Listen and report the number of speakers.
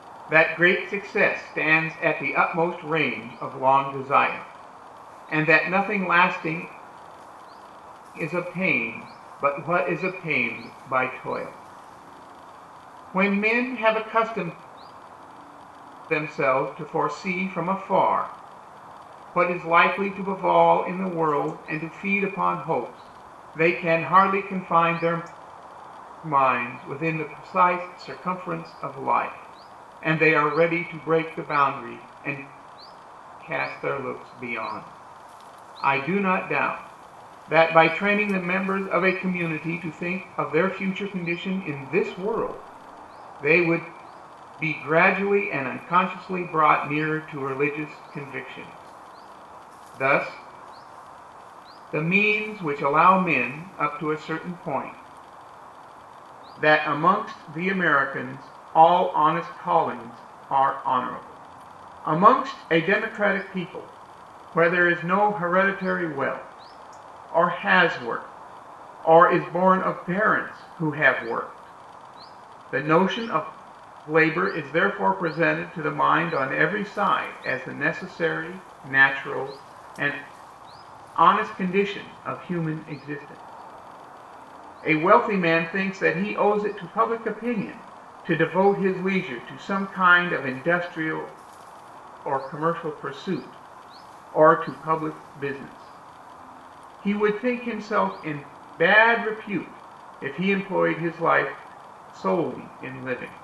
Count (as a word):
one